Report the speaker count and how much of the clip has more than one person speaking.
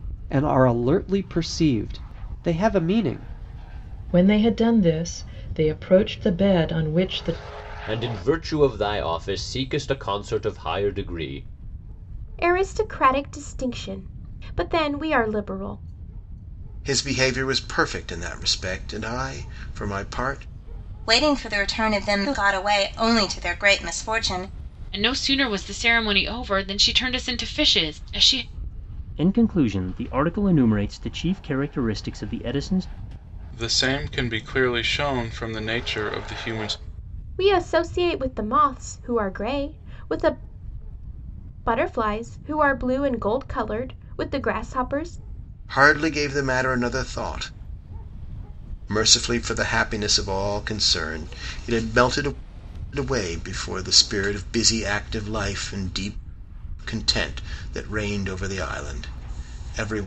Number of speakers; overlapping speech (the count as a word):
nine, no overlap